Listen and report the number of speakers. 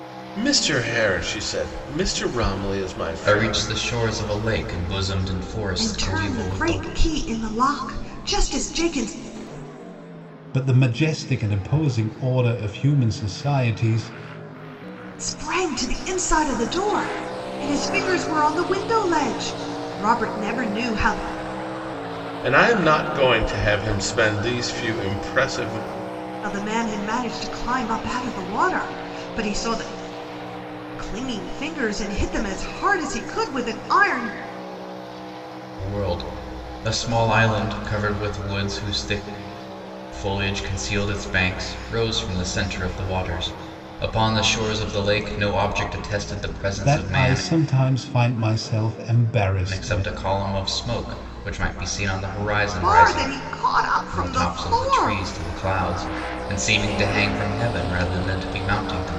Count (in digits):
4